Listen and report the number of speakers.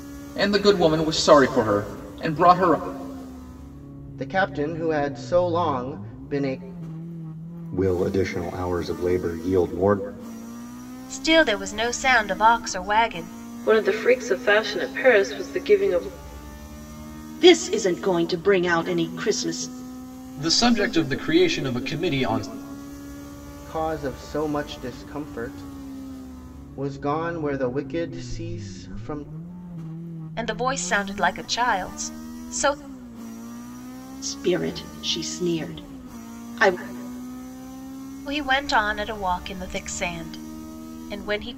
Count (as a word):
seven